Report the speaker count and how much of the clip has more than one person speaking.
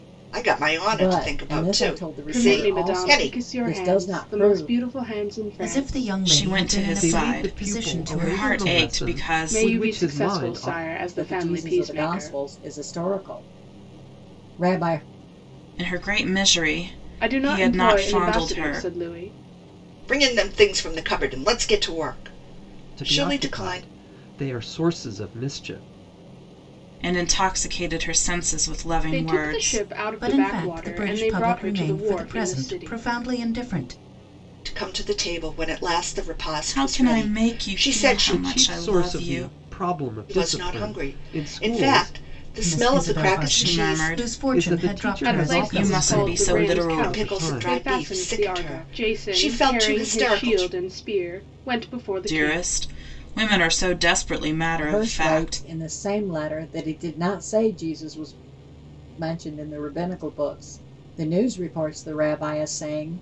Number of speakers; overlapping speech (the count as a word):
six, about 49%